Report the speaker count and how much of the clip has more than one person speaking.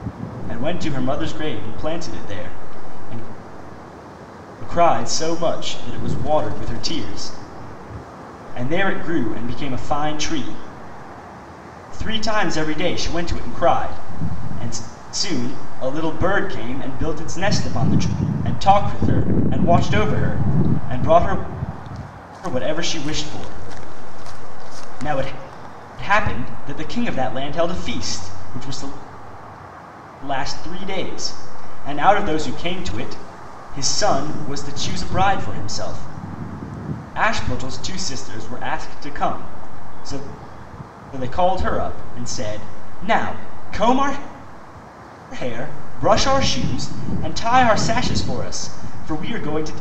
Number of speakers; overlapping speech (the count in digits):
1, no overlap